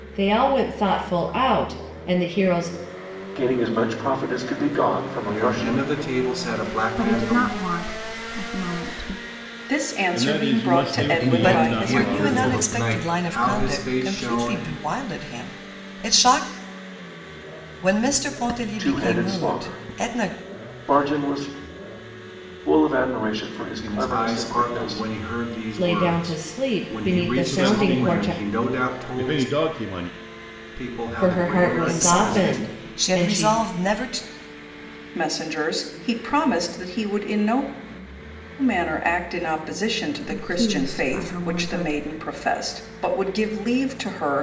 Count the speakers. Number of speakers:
eight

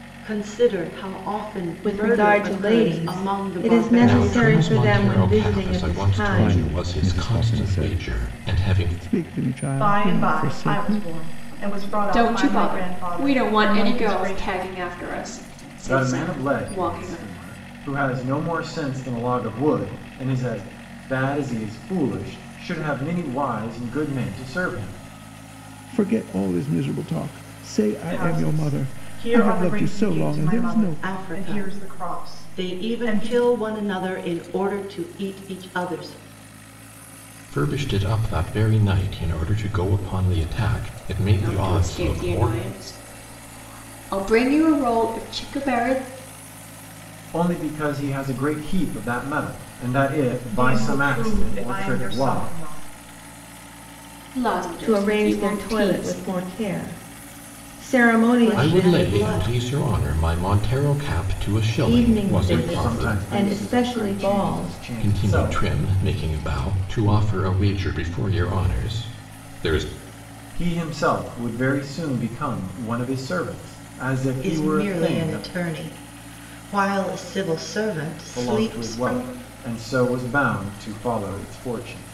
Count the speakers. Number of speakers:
seven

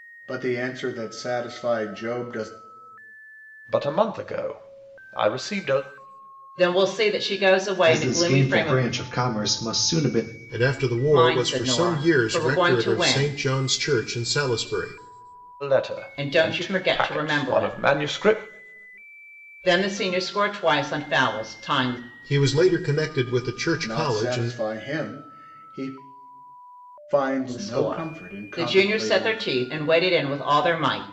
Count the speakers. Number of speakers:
five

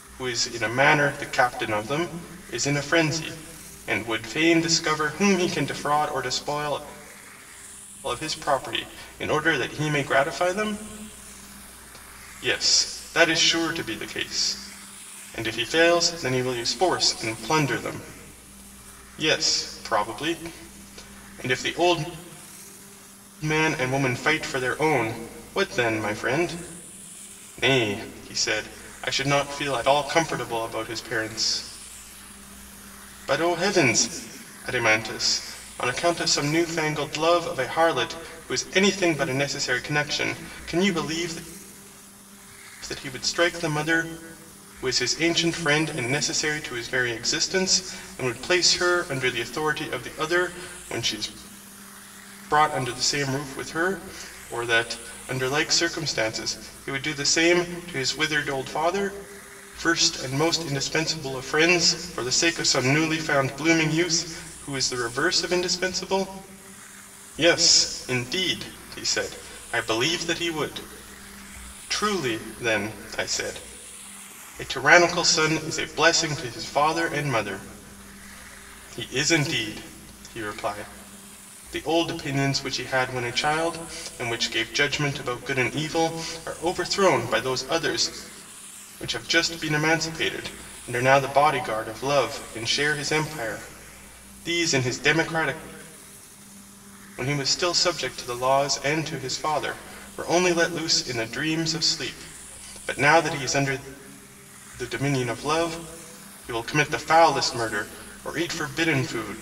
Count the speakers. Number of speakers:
one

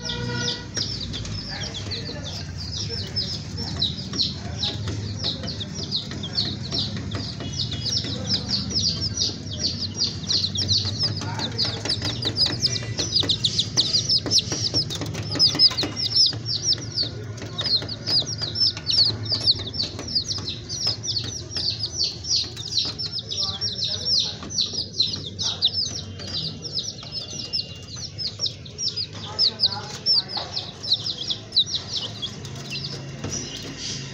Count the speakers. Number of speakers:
zero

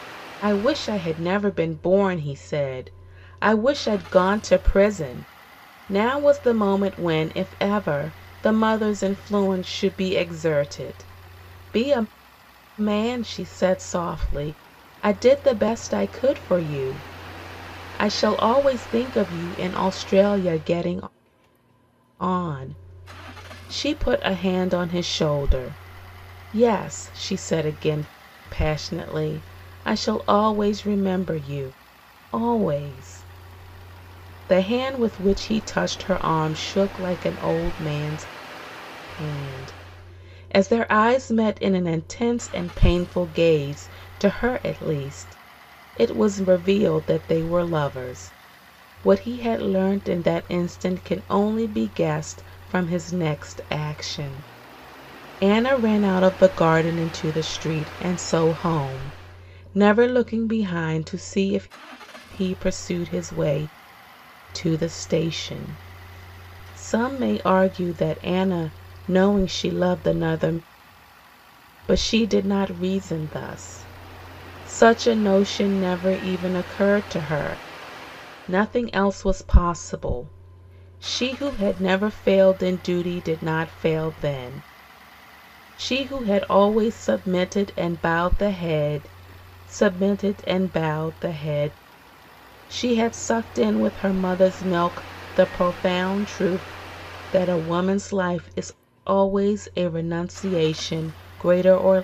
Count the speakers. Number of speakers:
one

